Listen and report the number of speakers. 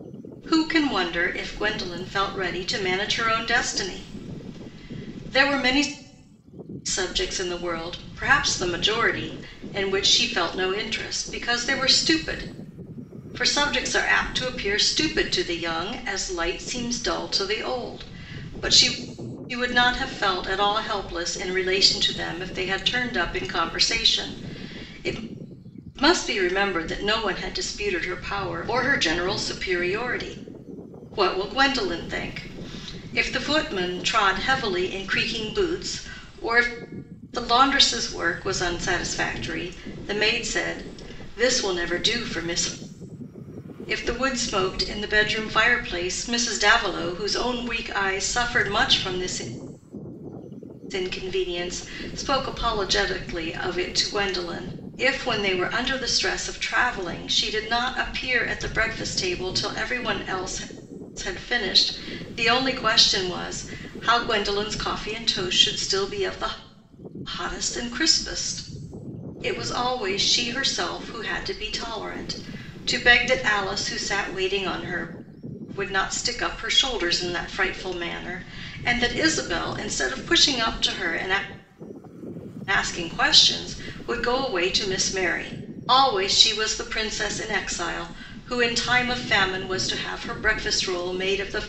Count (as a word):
one